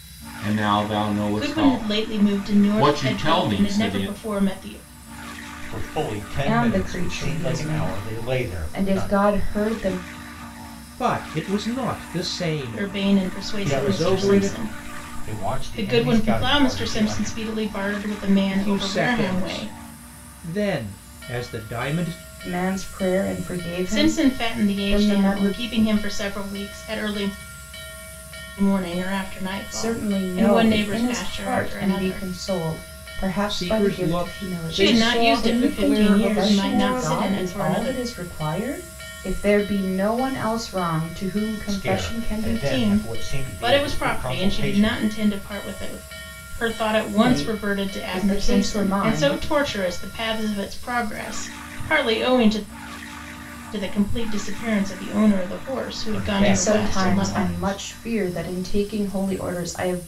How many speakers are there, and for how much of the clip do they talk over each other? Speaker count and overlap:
5, about 46%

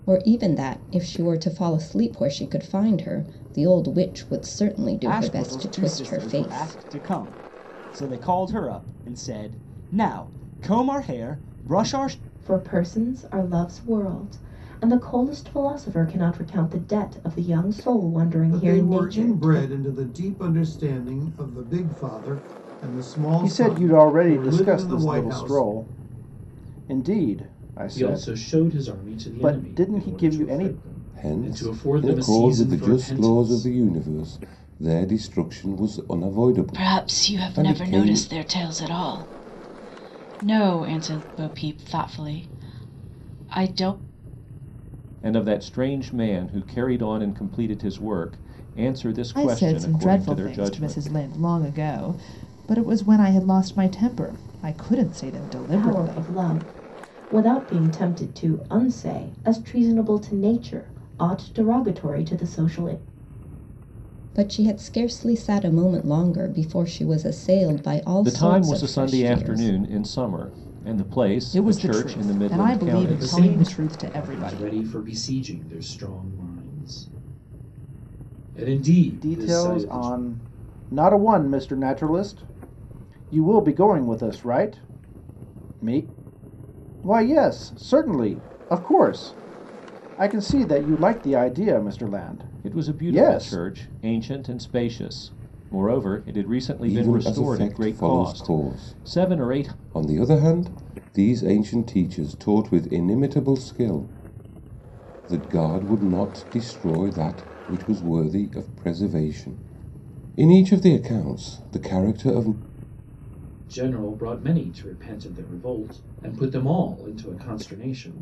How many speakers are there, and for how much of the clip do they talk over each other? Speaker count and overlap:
10, about 21%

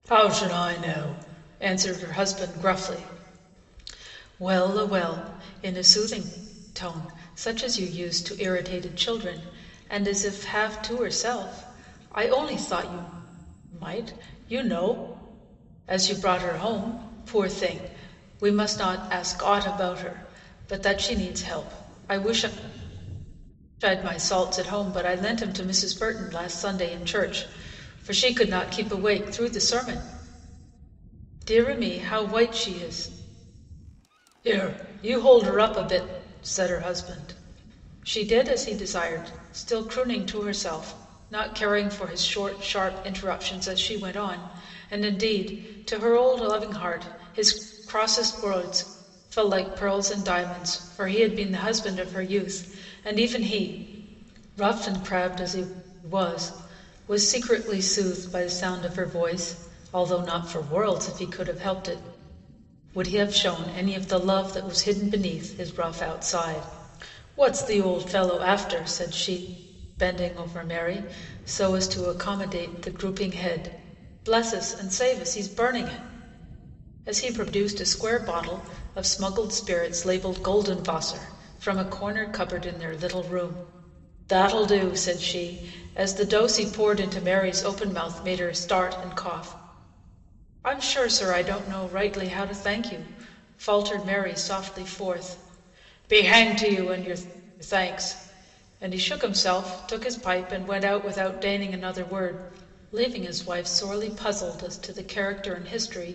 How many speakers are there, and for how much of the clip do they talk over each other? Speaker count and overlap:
1, no overlap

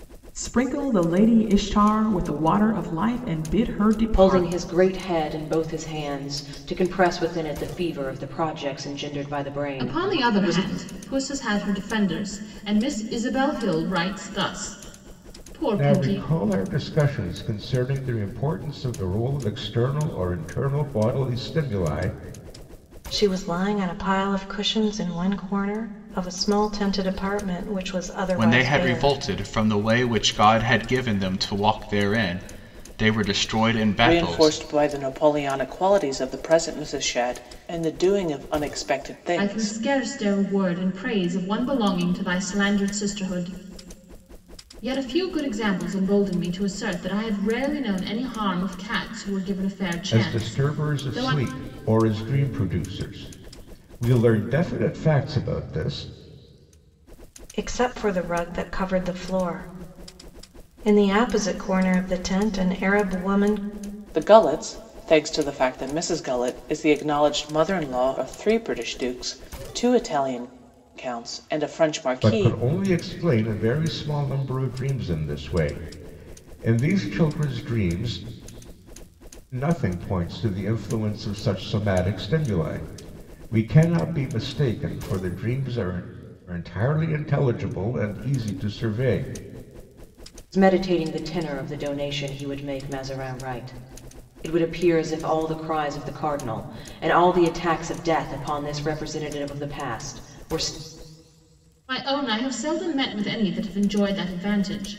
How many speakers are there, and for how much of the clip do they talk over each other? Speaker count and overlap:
7, about 5%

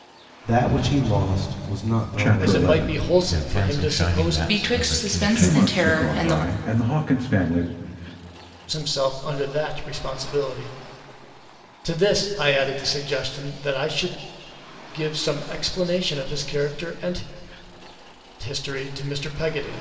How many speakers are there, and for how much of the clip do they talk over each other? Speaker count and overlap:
5, about 21%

